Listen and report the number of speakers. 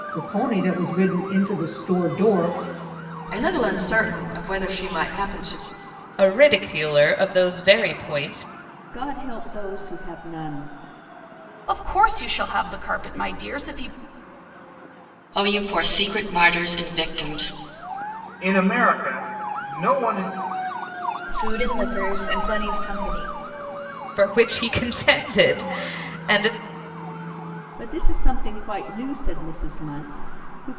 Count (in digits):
8